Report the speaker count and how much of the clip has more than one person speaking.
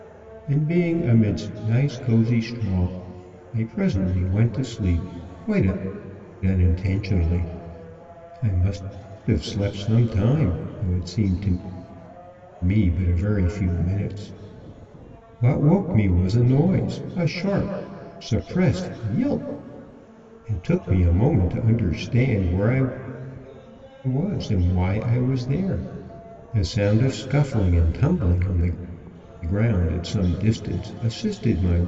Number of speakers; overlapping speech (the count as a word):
one, no overlap